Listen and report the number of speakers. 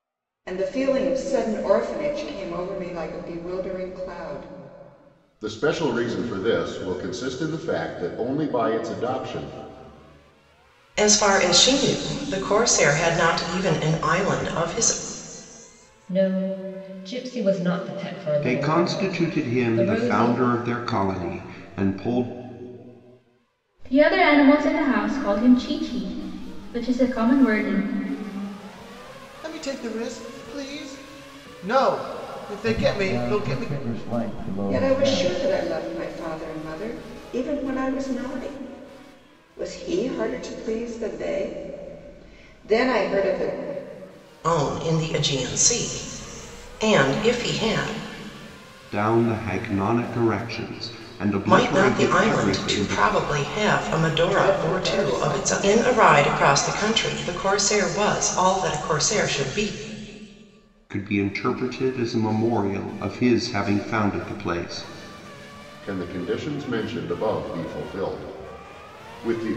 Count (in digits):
8